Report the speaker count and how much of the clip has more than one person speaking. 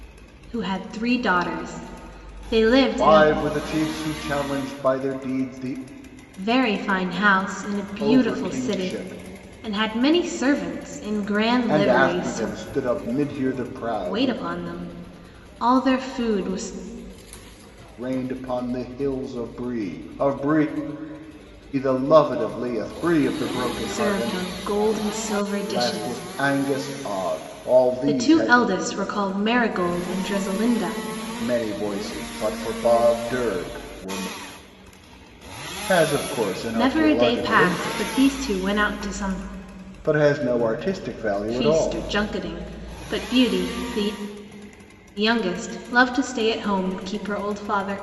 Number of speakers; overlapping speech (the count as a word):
two, about 13%